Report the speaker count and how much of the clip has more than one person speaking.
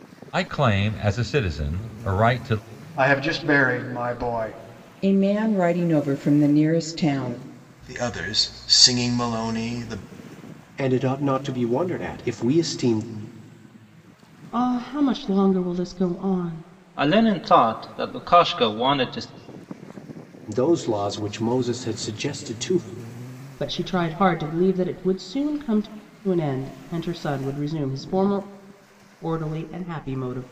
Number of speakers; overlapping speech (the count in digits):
7, no overlap